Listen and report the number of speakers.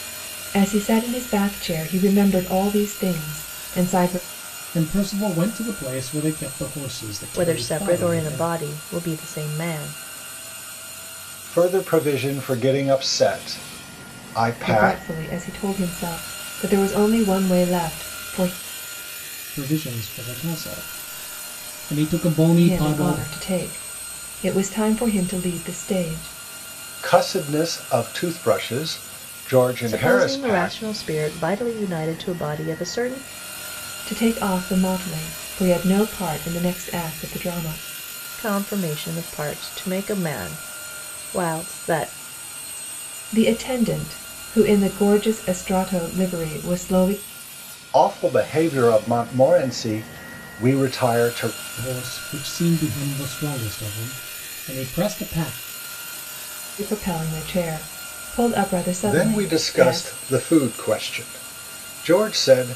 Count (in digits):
4